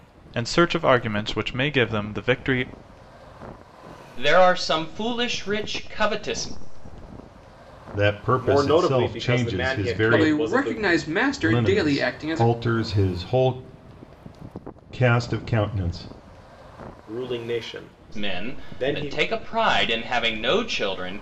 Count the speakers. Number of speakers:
5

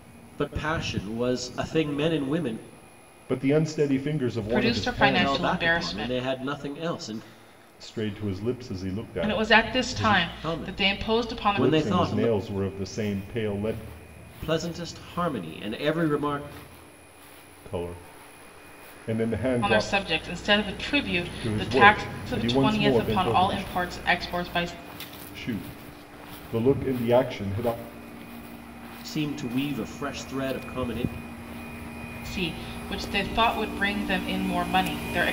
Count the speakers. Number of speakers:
3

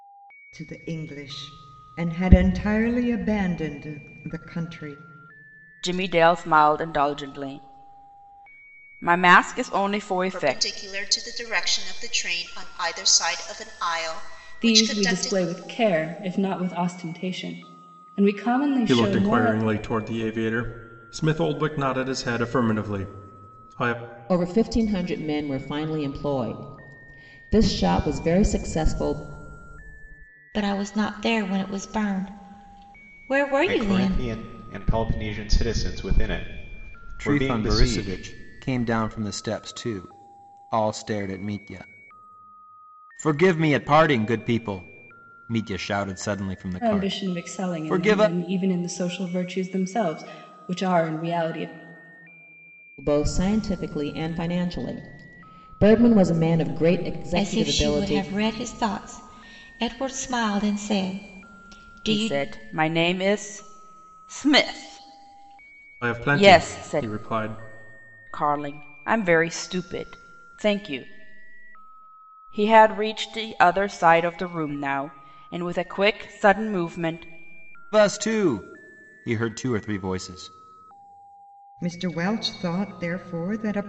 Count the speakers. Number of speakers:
9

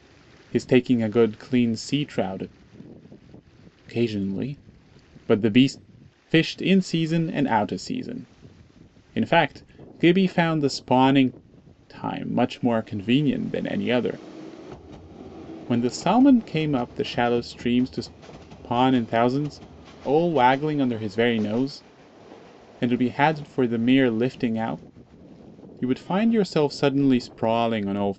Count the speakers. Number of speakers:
1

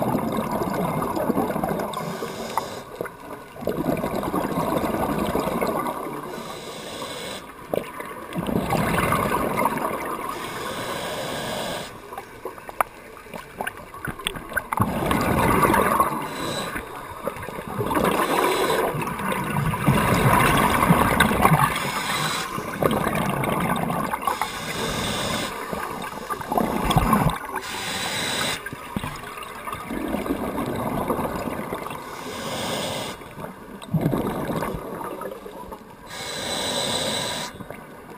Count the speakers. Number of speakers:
0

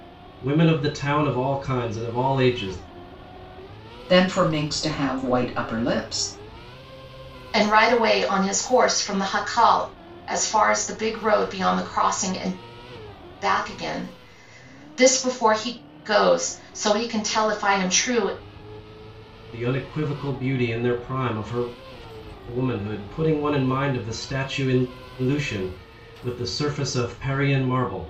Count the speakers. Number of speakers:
3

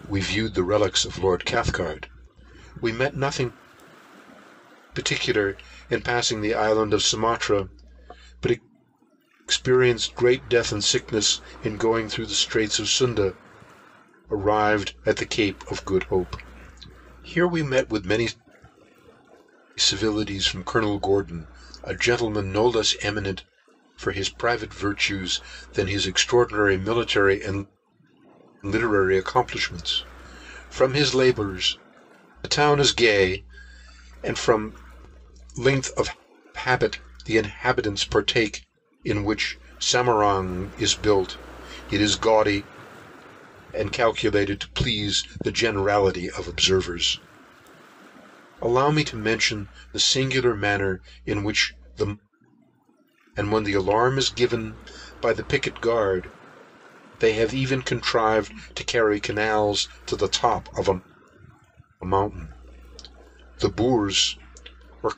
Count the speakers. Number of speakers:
1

